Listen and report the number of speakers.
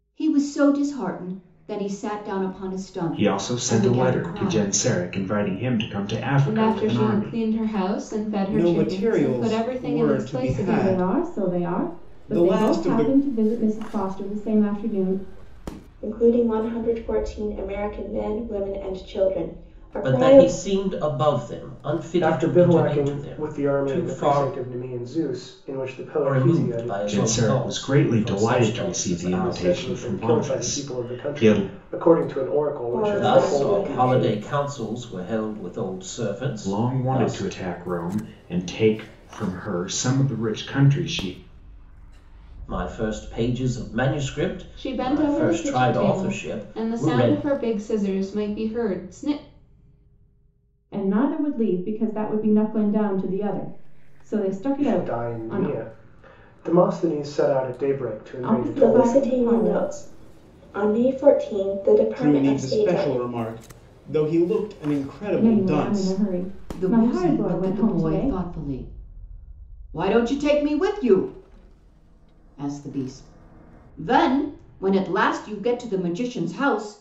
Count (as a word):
eight